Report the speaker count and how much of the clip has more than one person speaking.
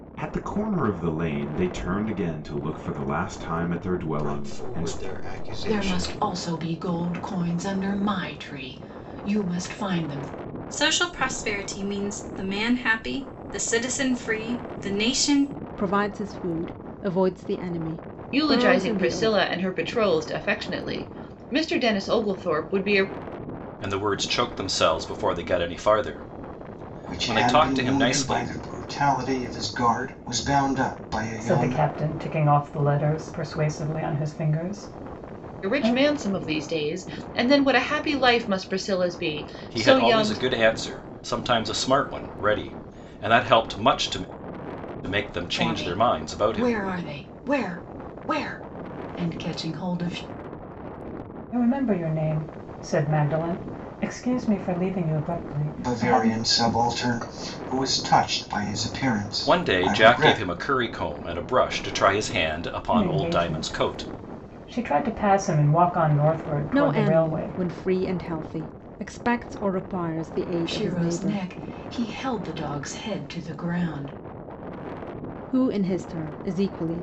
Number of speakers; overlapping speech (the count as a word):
nine, about 15%